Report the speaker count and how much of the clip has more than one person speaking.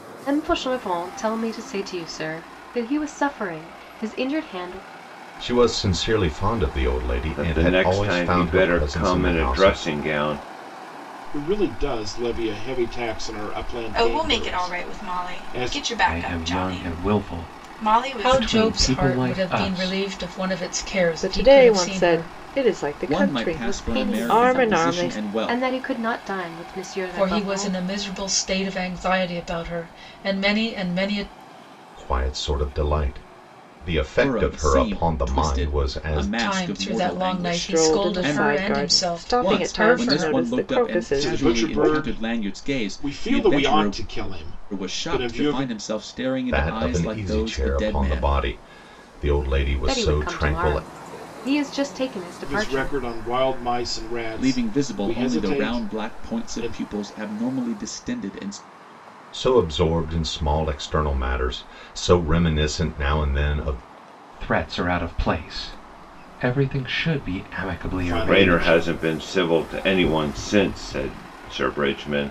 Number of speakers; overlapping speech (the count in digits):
9, about 42%